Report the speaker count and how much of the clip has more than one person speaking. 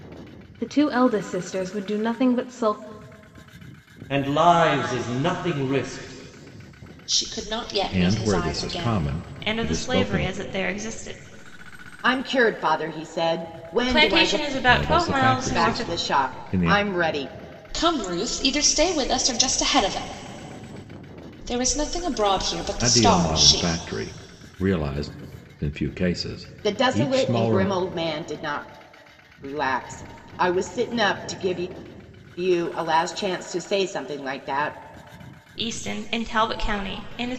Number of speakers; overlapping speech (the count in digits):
6, about 18%